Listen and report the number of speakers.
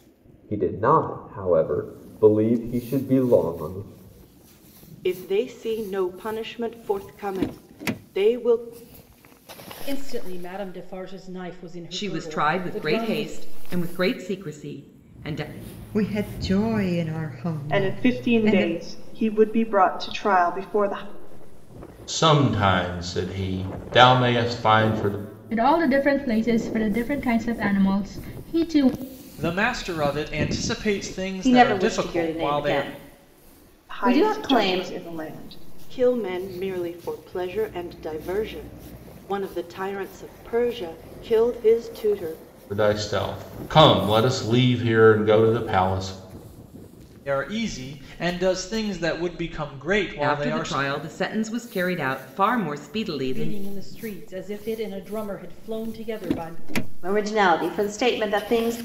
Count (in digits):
10